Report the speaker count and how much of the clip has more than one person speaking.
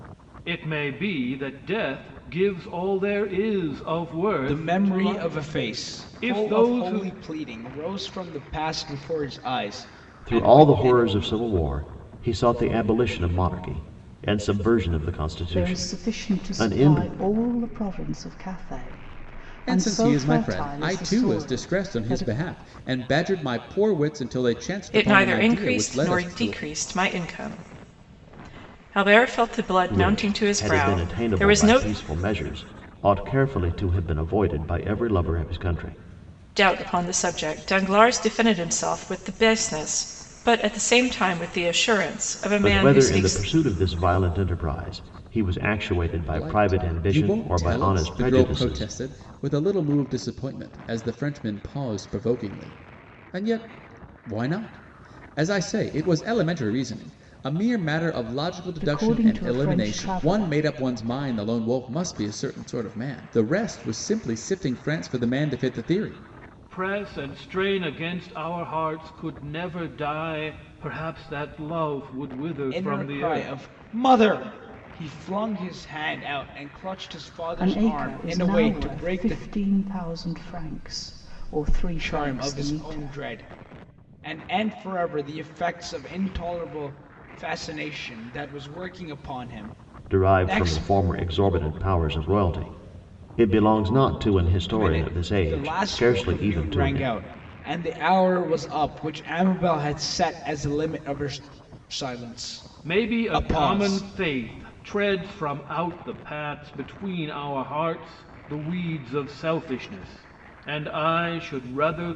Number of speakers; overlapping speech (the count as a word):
six, about 22%